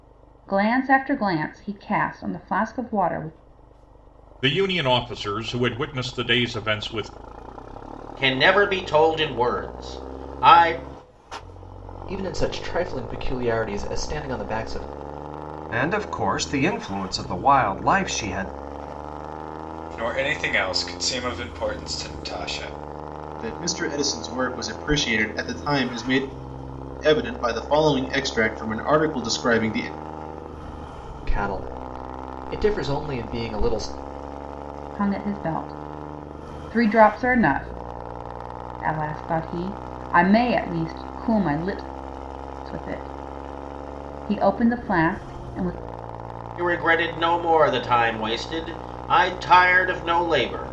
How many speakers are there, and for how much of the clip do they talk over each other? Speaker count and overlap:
seven, no overlap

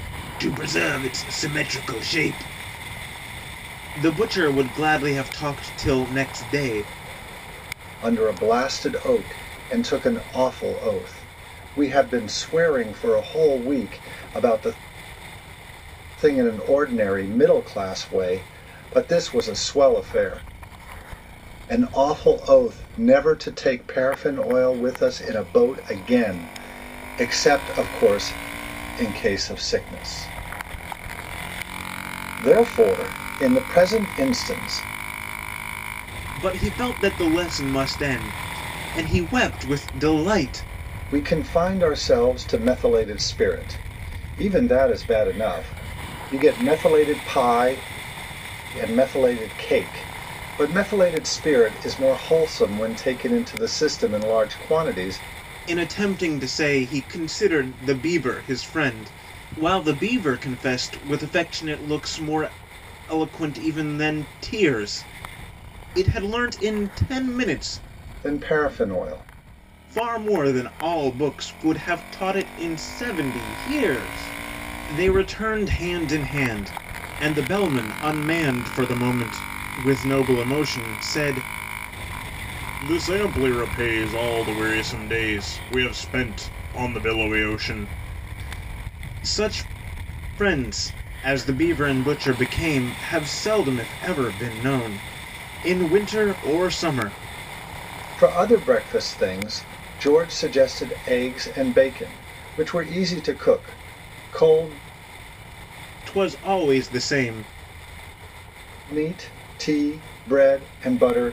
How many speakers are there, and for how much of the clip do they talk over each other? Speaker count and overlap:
two, no overlap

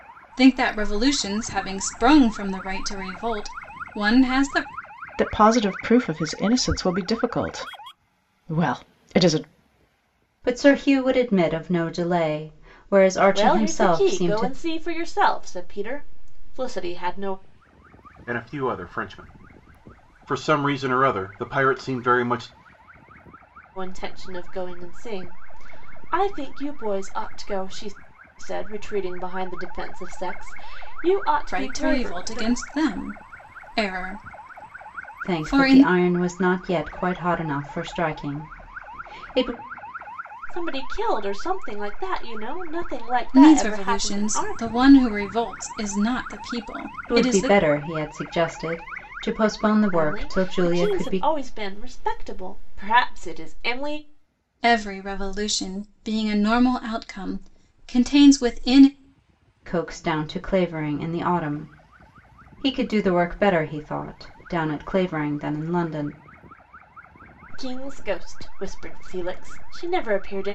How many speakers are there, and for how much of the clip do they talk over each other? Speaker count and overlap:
five, about 9%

